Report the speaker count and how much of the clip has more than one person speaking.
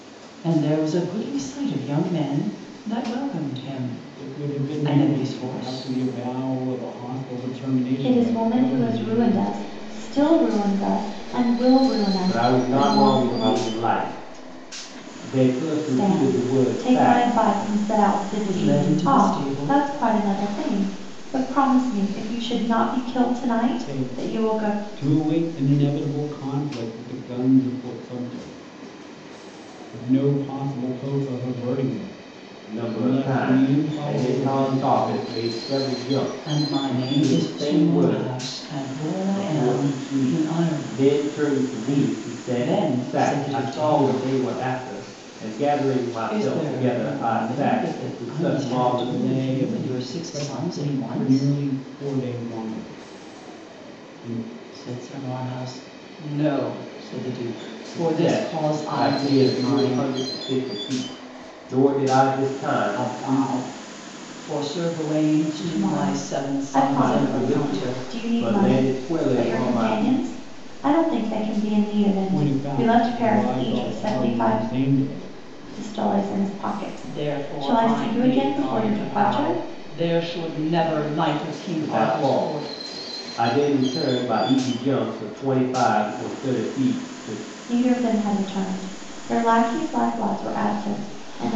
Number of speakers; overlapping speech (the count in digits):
4, about 40%